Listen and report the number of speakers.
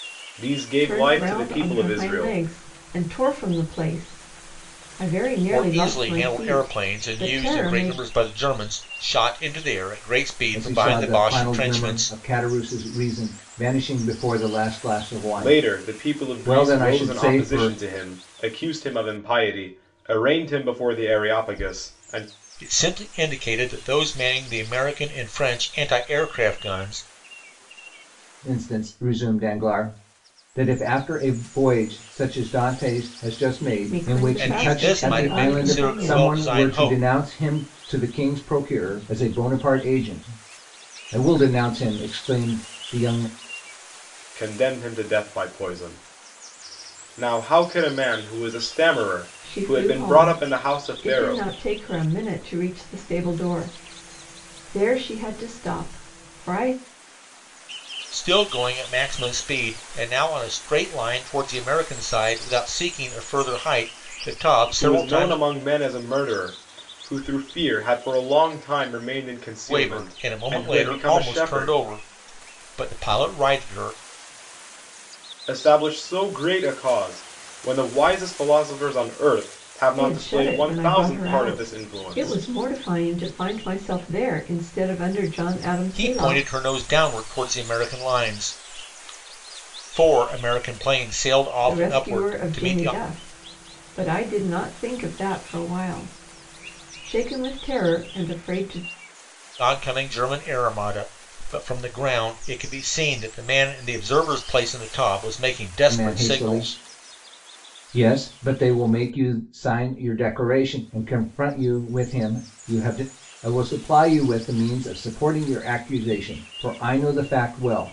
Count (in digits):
4